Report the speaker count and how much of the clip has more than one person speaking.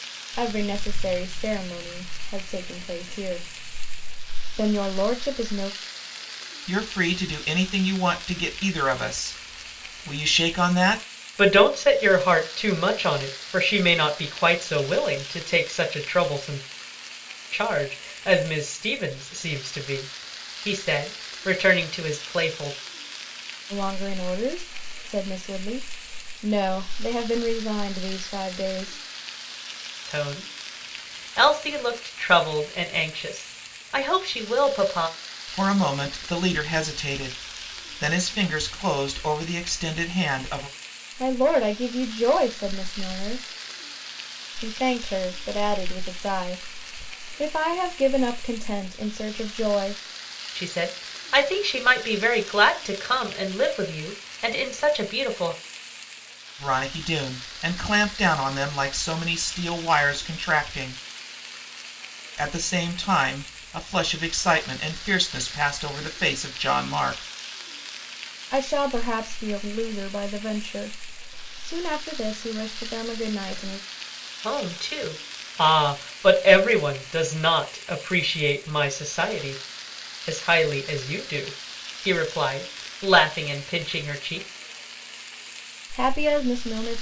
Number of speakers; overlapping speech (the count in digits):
3, no overlap